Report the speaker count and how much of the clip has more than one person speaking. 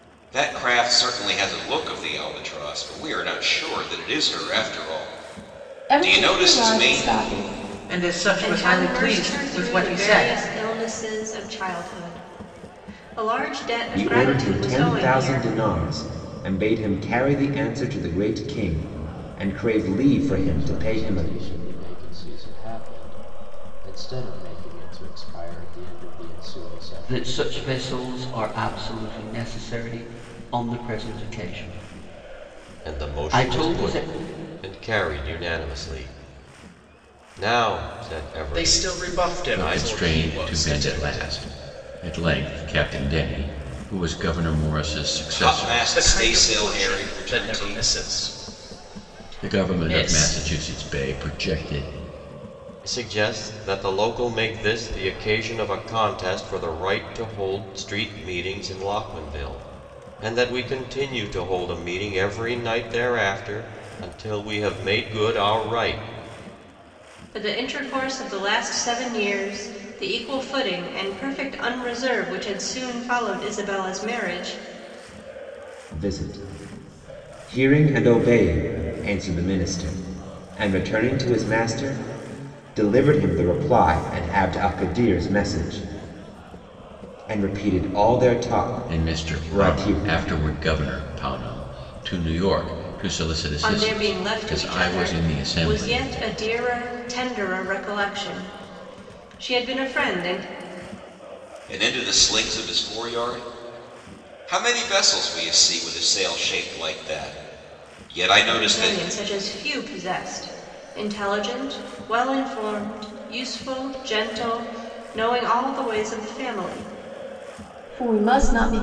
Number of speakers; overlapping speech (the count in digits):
10, about 15%